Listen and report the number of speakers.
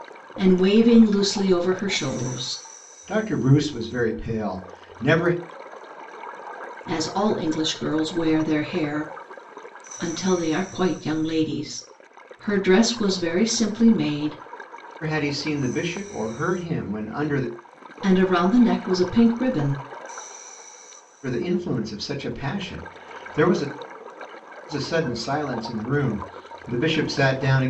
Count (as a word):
two